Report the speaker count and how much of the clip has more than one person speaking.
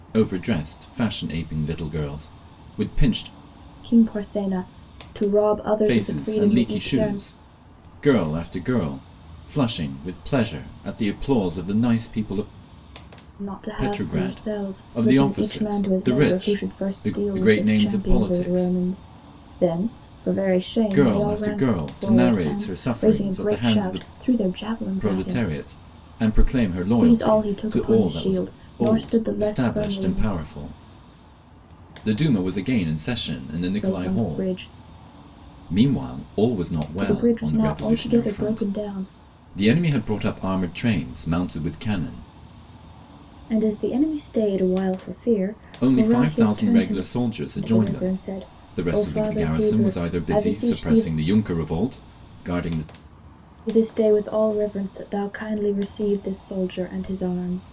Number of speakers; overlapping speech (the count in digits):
2, about 35%